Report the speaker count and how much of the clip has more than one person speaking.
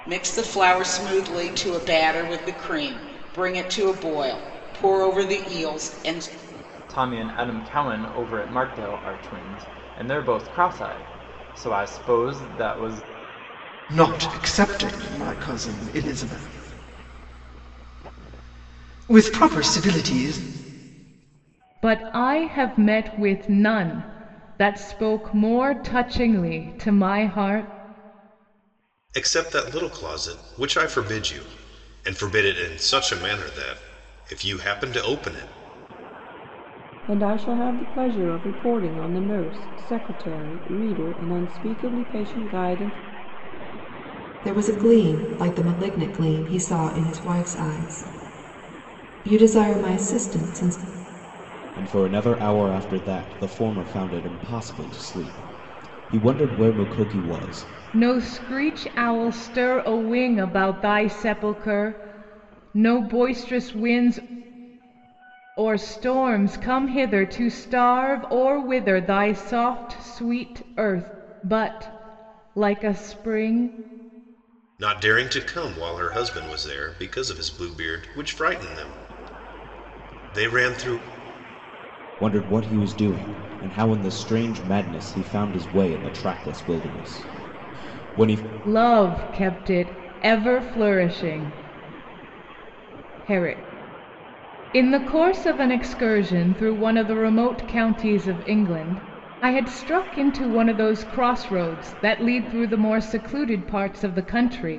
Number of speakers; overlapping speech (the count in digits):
8, no overlap